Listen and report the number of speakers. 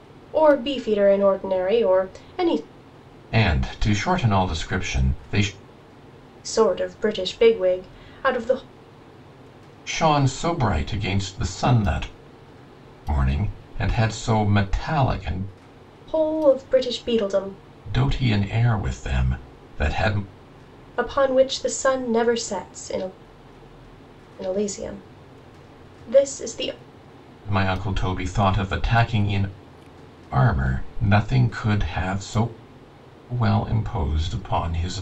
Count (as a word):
two